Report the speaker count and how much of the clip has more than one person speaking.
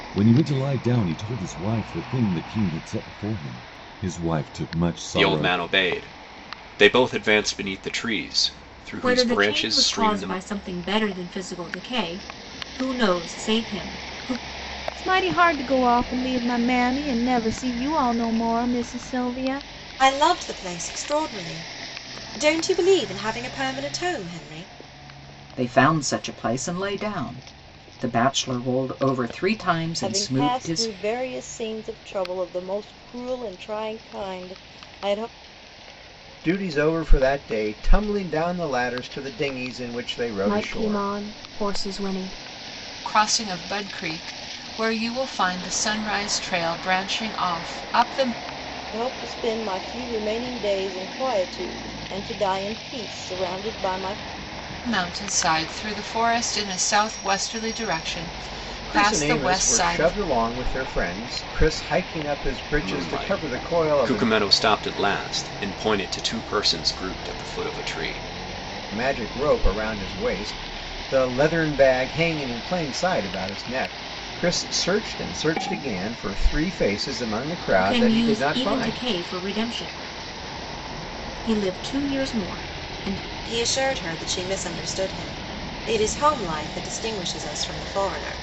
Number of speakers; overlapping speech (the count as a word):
ten, about 9%